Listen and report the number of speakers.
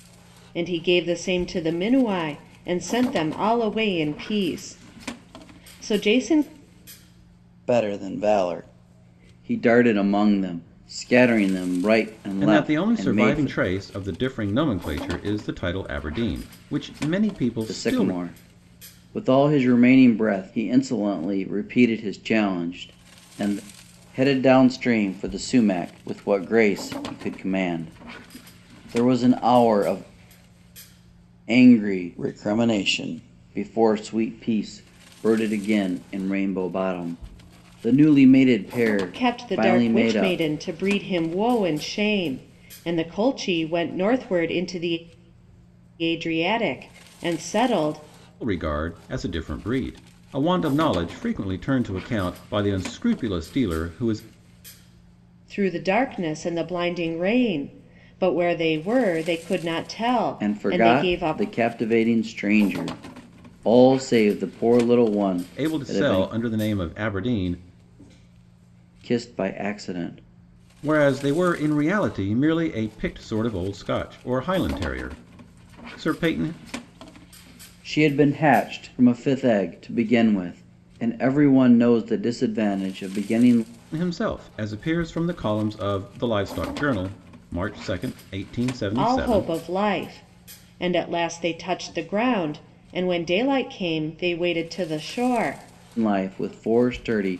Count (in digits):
3